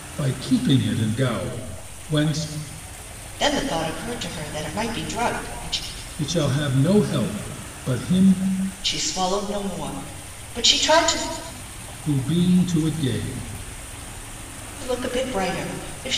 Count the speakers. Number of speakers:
2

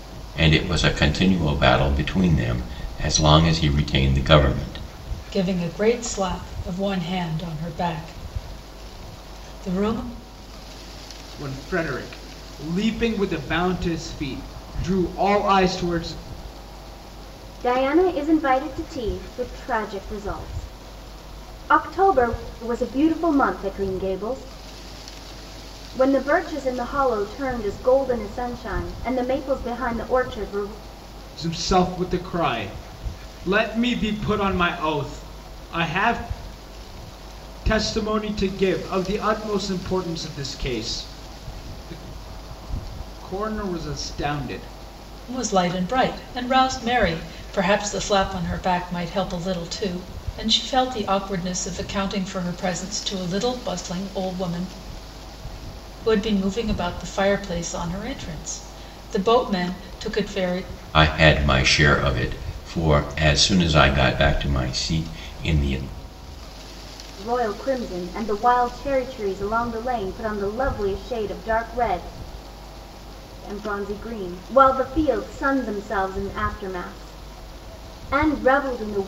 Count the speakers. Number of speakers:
4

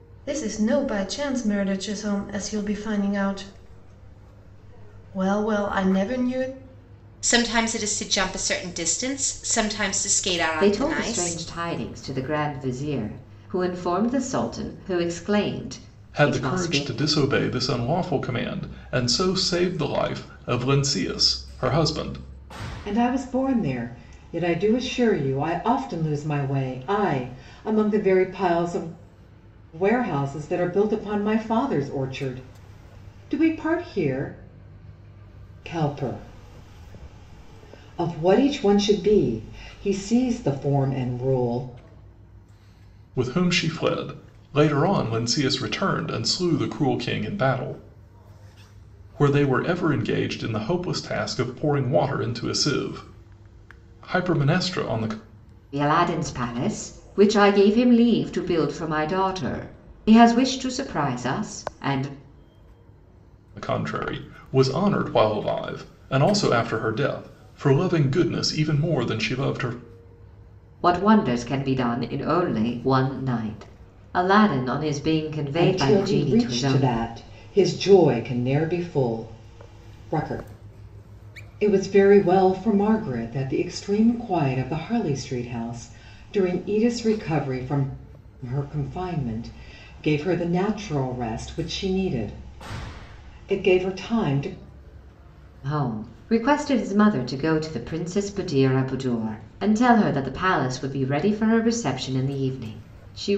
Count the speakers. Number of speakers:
5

